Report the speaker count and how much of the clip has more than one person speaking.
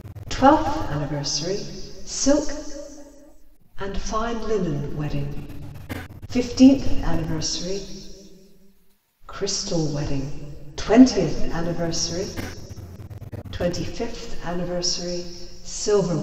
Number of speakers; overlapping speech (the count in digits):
1, no overlap